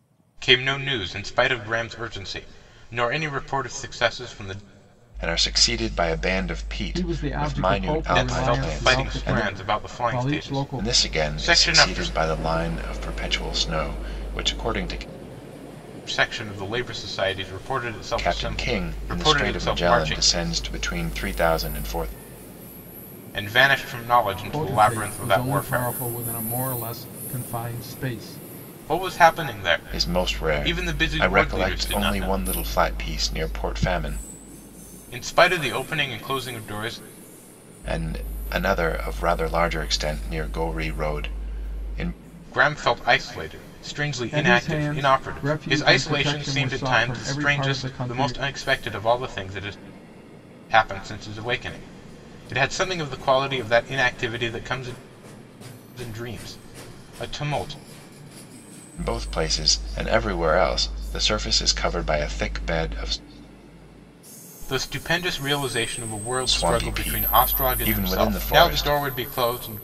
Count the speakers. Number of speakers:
3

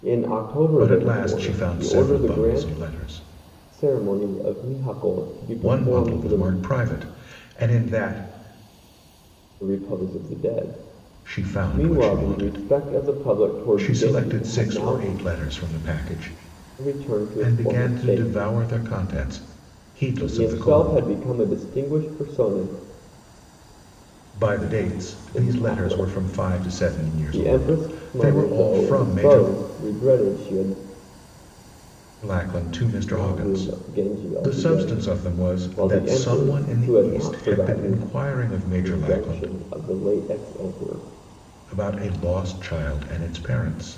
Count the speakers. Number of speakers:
2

